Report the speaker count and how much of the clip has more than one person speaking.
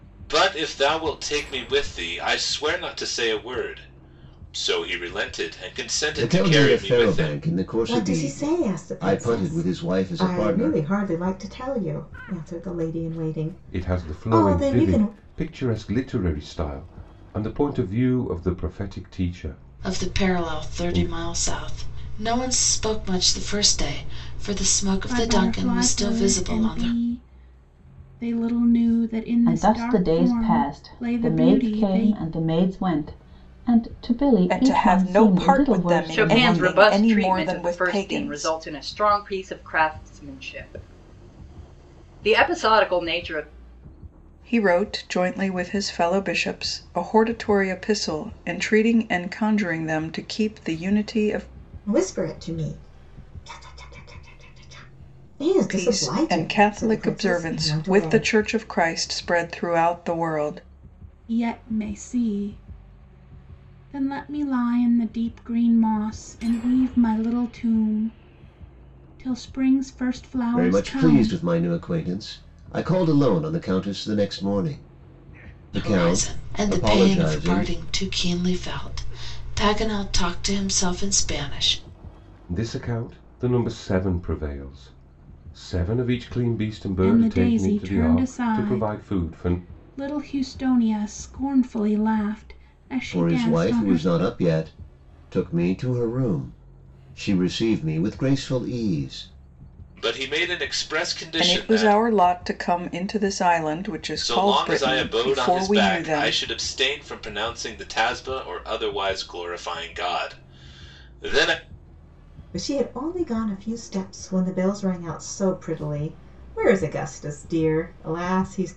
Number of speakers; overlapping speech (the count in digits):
9, about 23%